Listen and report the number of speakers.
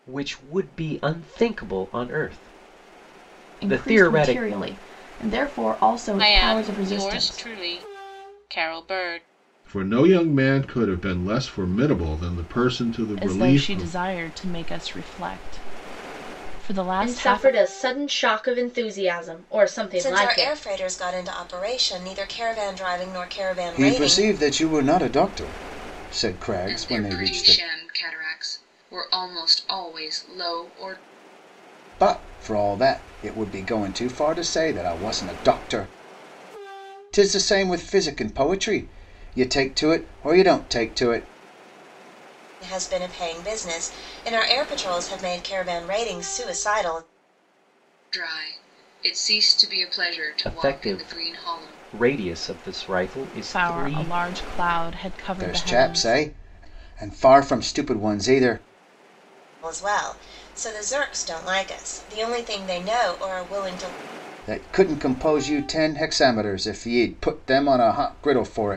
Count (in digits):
9